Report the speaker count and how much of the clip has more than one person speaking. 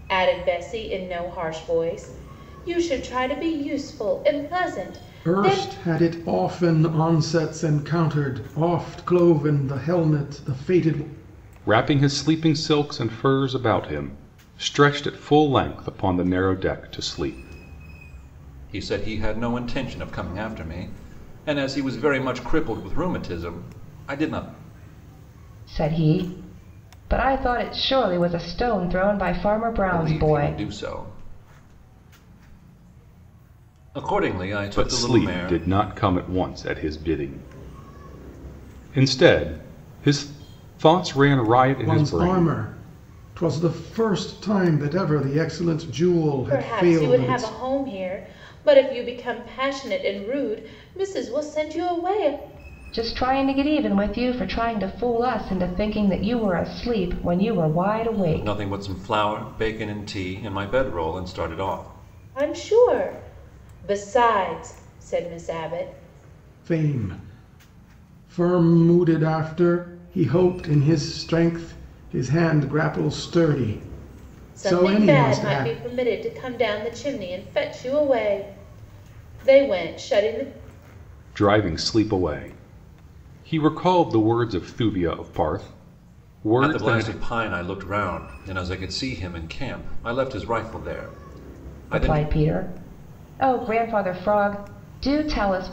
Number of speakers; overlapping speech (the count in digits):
5, about 7%